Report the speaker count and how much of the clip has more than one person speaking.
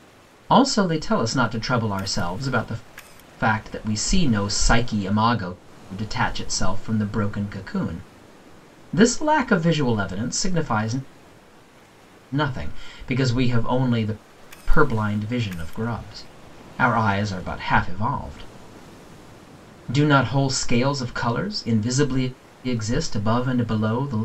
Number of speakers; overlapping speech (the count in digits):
1, no overlap